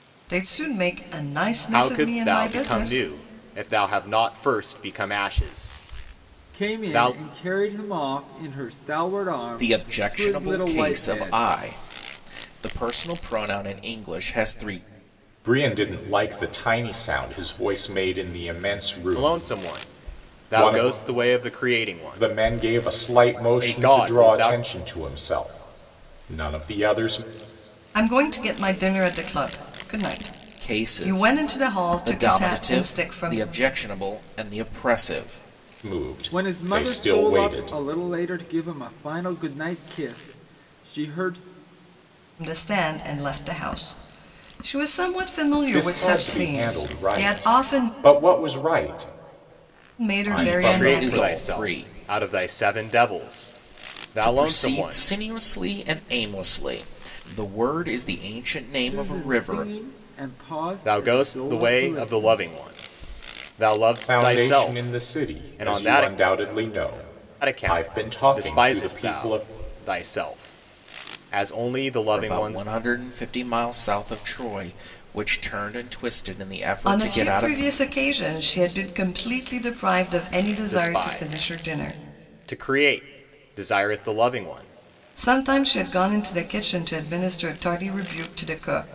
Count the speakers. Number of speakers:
5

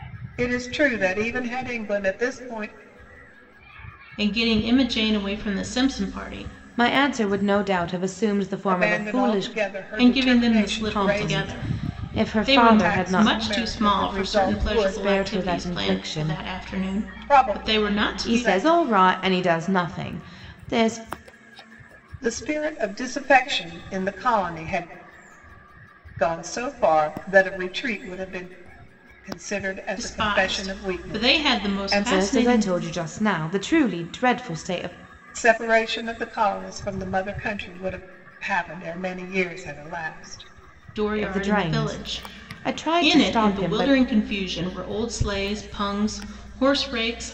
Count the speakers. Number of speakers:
3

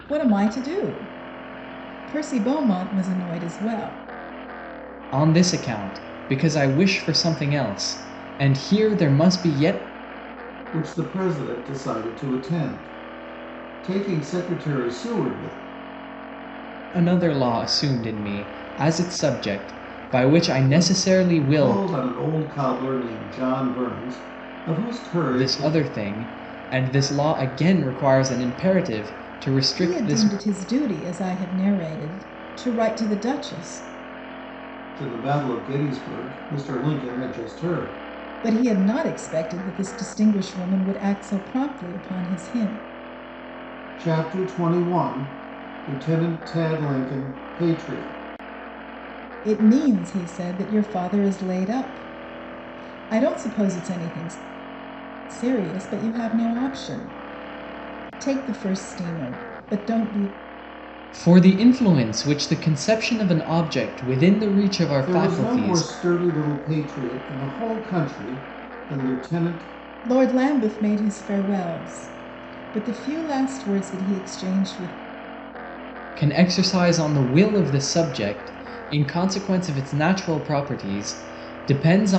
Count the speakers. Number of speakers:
3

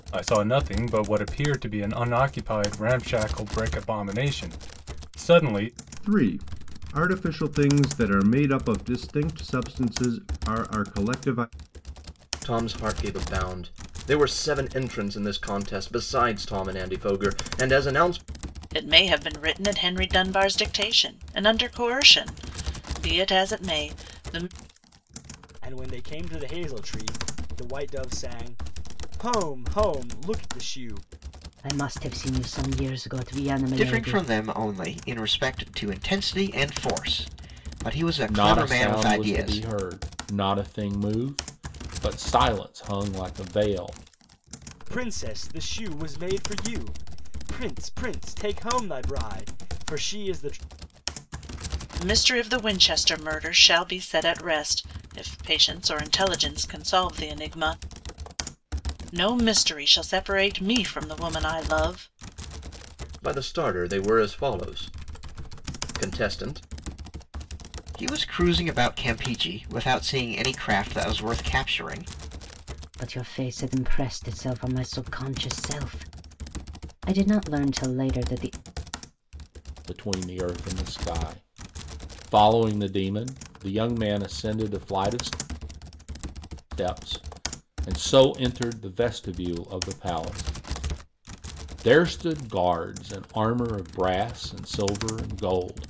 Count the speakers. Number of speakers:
8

